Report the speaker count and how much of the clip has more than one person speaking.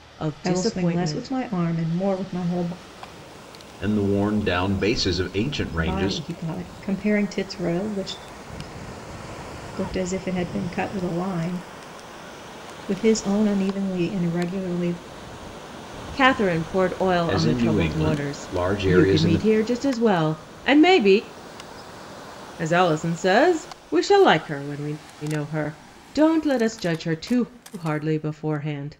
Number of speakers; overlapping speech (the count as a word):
three, about 11%